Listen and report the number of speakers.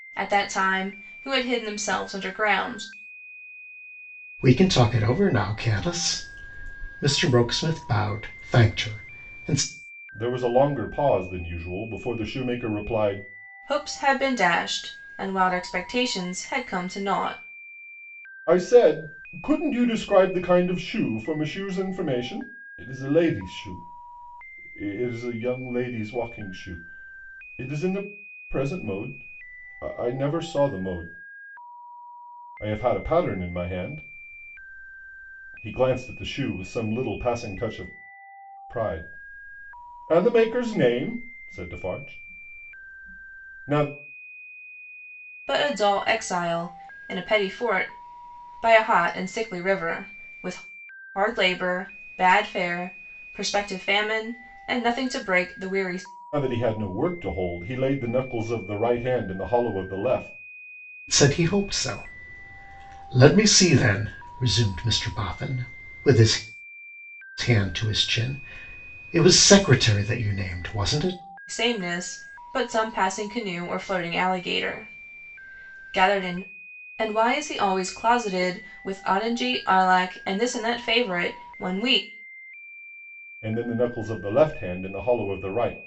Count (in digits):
3